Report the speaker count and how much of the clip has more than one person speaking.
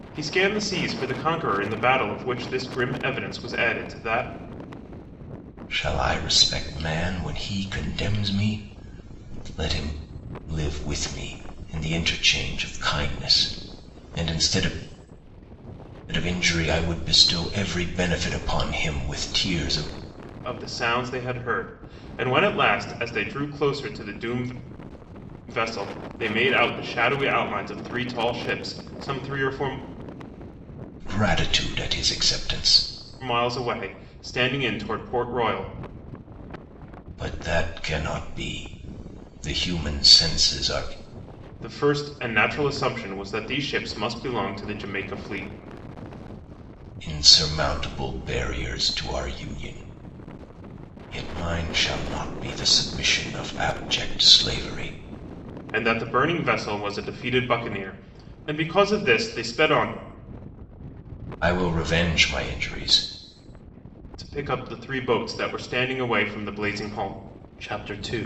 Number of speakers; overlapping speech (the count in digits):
2, no overlap